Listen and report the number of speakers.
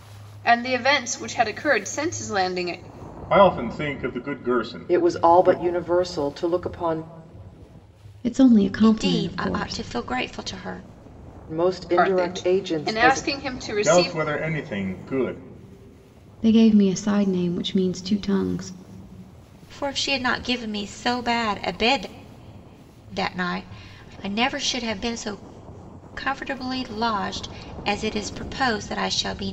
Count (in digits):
5